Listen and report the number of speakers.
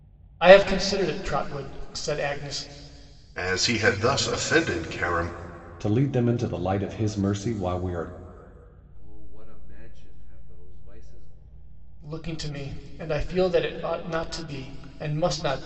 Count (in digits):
4